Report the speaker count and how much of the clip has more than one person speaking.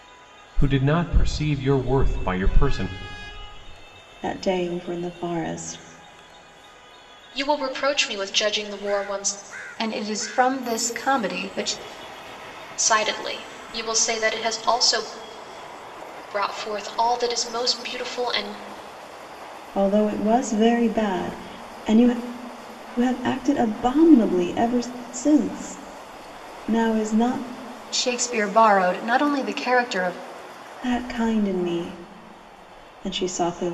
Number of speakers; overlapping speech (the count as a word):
four, no overlap